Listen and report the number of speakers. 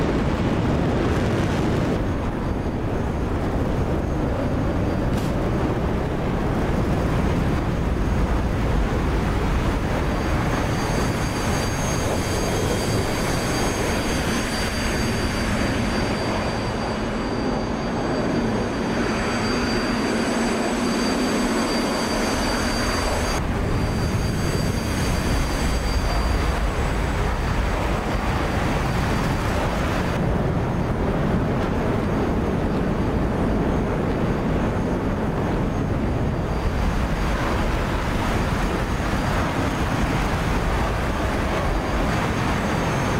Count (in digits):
0